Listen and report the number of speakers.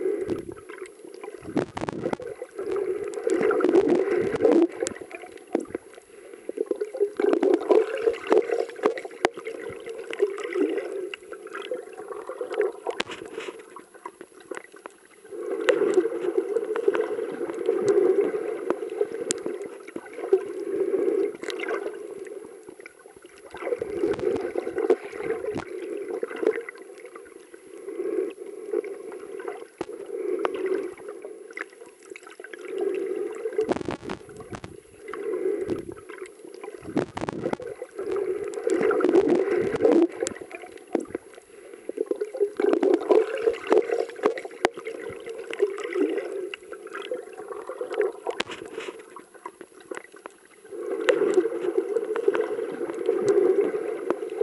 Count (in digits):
0